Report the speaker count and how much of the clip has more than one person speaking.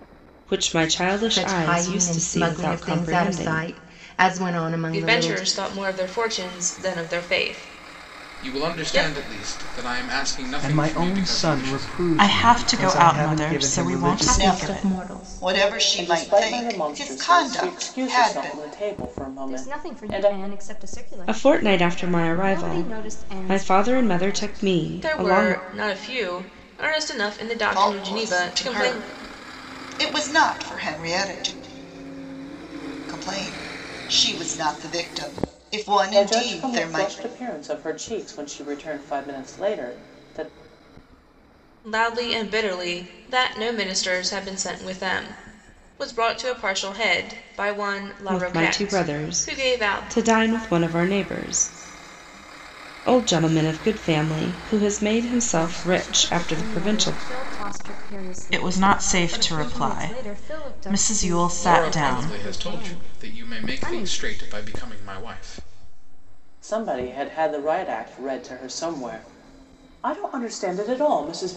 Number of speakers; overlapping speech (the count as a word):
ten, about 38%